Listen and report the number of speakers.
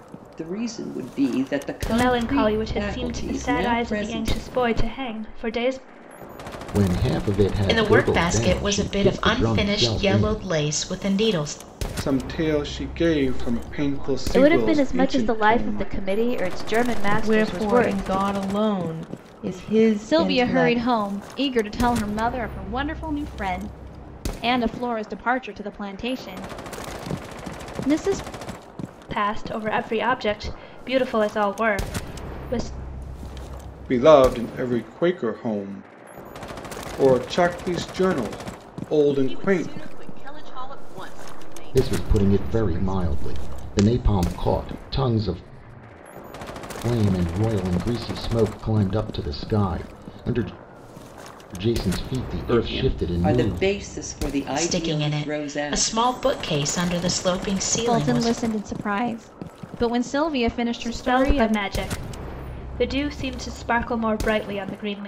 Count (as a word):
nine